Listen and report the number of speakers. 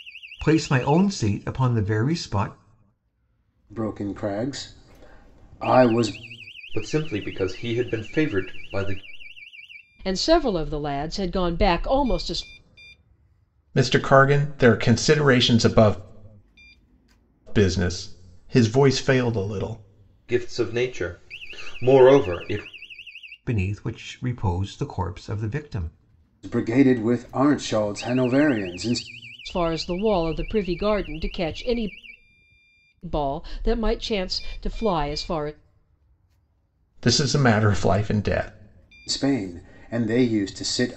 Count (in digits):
5